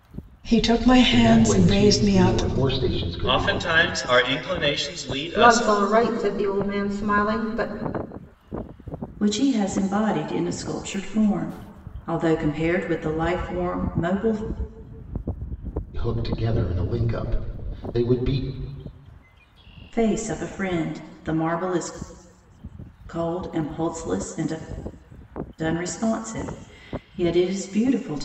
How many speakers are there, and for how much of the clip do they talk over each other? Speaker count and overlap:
5, about 7%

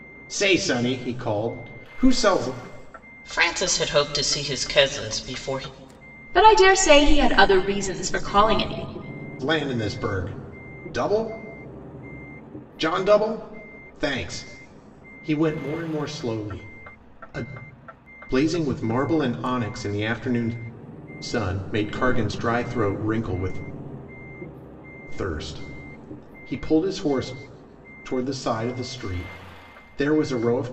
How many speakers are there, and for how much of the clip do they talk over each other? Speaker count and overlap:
3, no overlap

